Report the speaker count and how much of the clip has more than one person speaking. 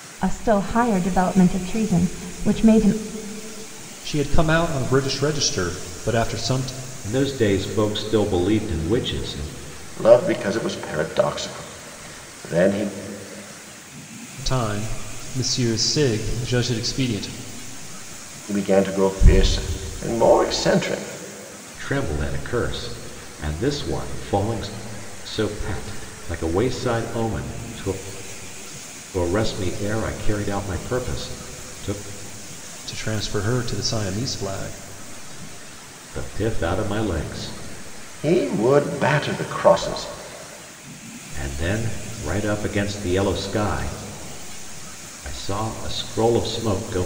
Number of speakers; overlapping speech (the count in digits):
4, no overlap